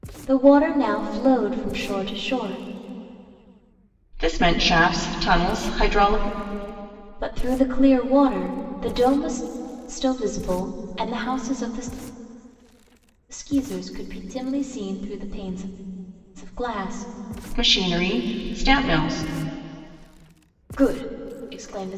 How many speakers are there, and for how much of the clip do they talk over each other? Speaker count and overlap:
2, no overlap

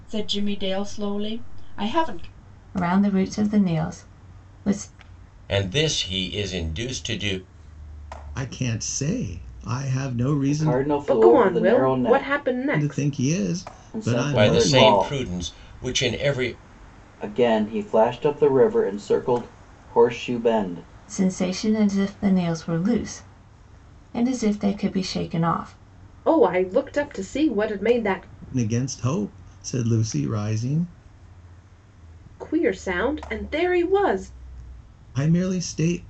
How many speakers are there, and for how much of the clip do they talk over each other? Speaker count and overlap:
6, about 9%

